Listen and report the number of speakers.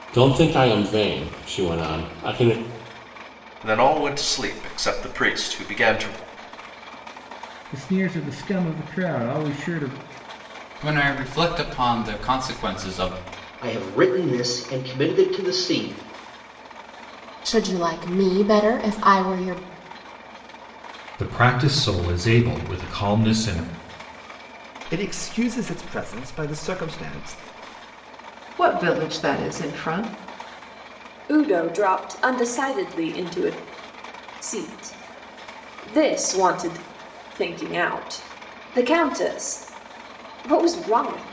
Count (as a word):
ten